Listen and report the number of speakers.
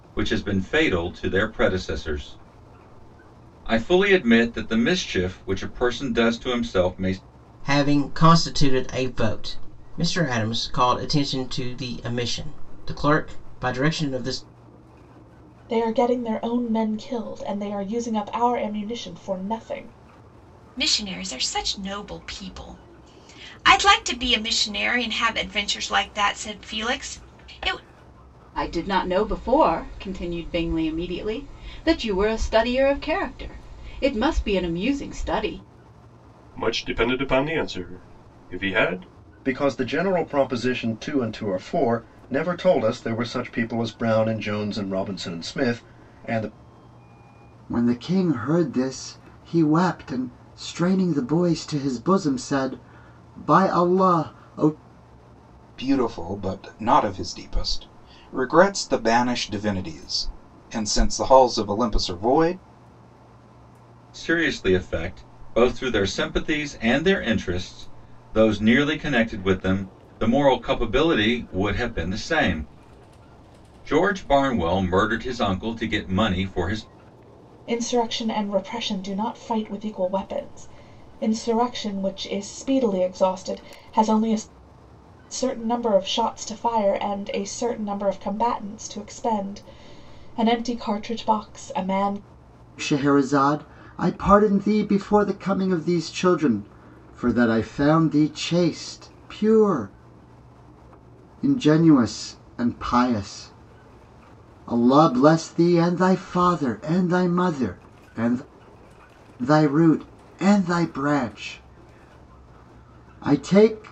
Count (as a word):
nine